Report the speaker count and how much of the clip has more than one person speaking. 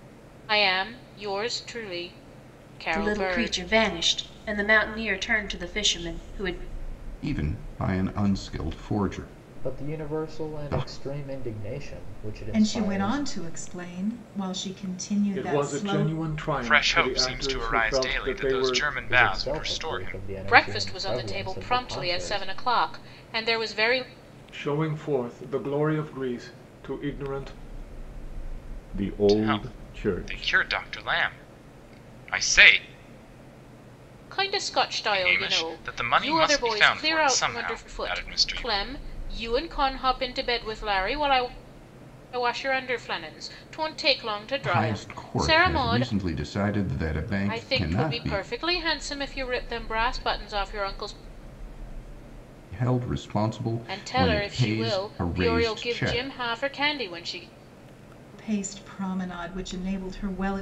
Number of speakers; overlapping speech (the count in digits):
7, about 31%